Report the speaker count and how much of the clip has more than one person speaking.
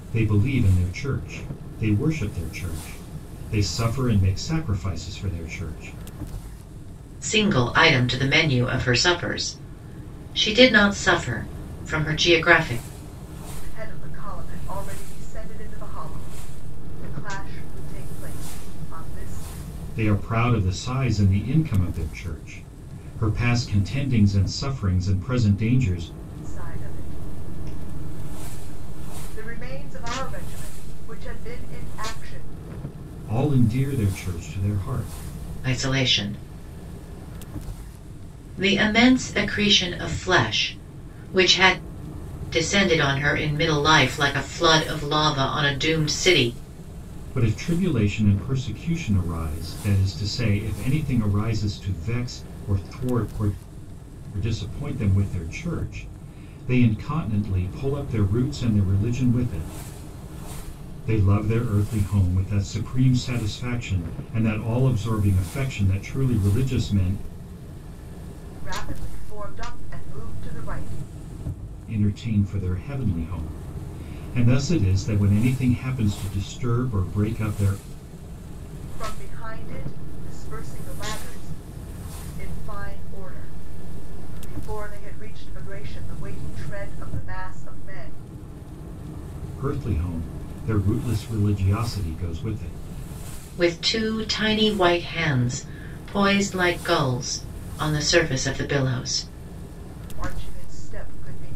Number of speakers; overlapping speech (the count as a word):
three, no overlap